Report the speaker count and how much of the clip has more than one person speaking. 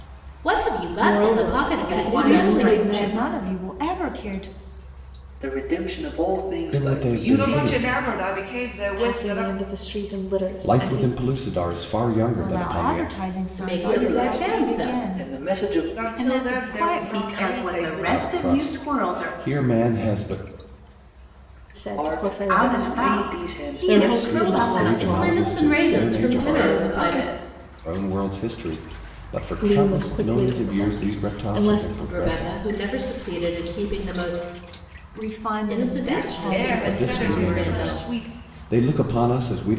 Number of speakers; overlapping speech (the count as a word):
seven, about 56%